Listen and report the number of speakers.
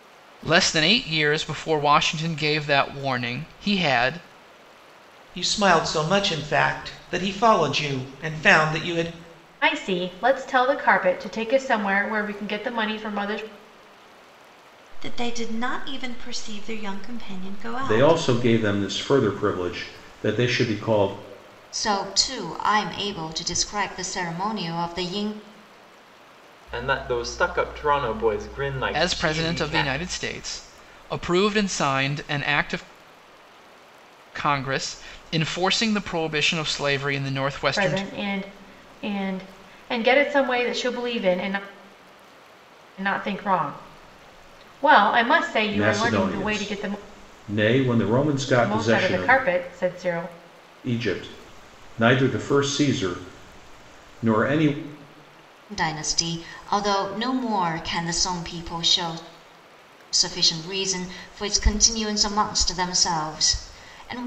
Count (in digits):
7